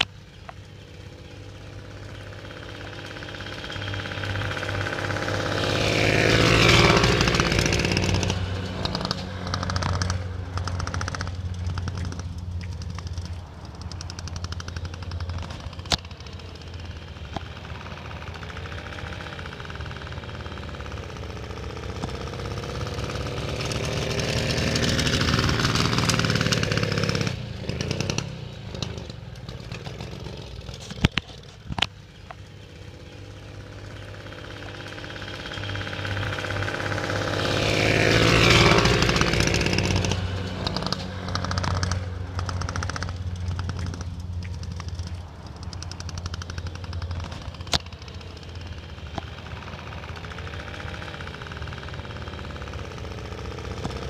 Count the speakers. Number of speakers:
0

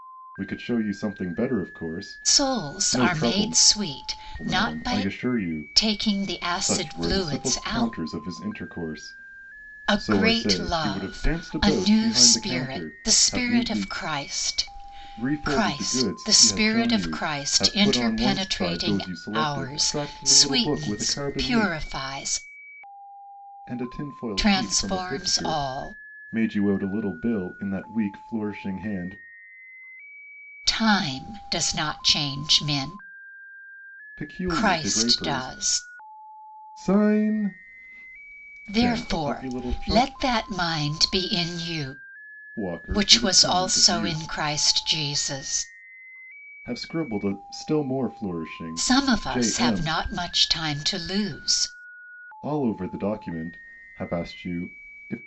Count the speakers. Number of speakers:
2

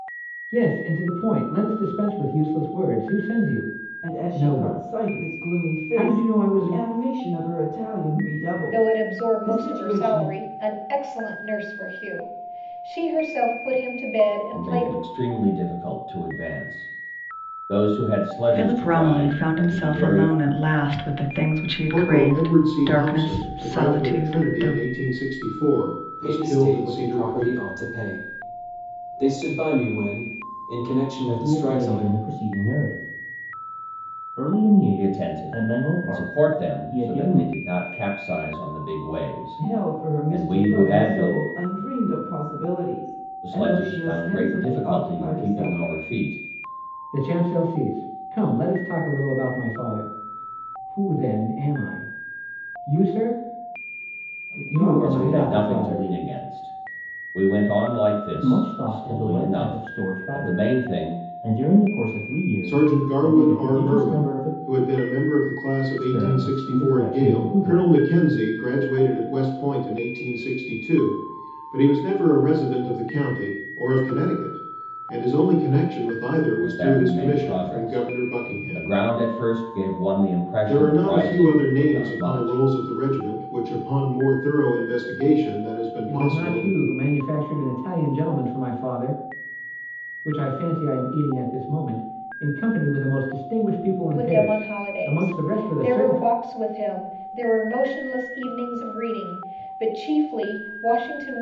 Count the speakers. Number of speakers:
8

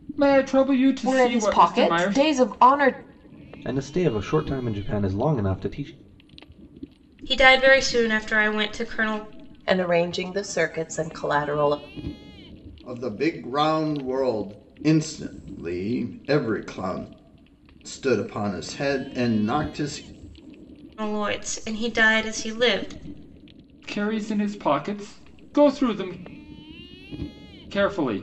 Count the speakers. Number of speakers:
6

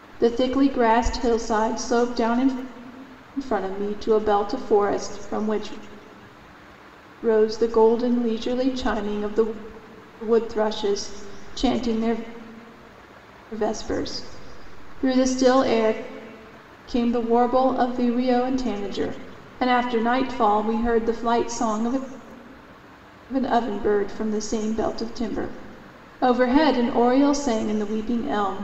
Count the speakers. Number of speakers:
1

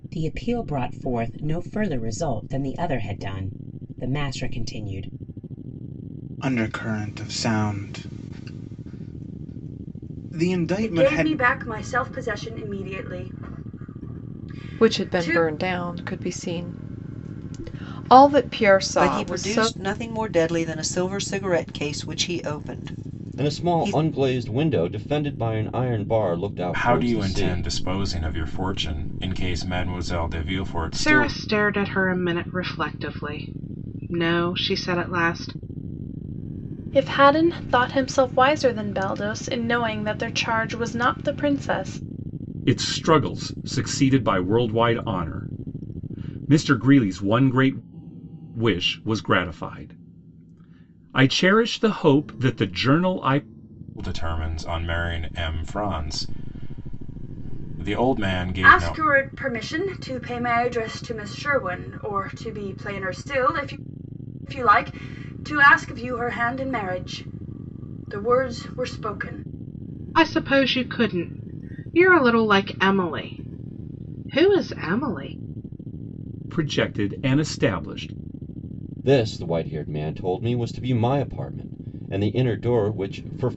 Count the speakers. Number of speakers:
10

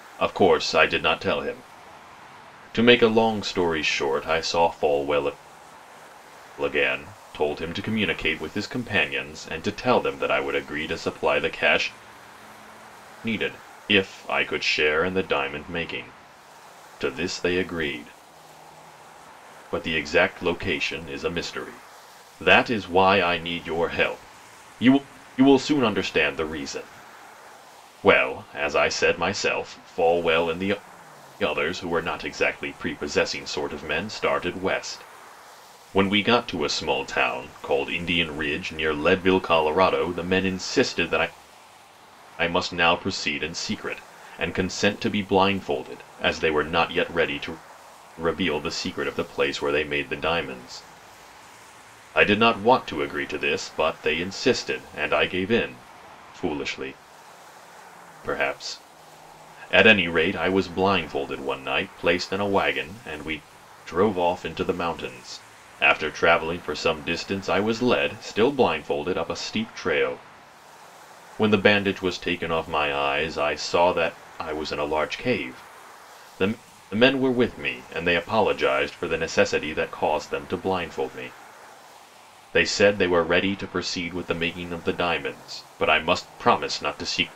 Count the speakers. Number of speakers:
1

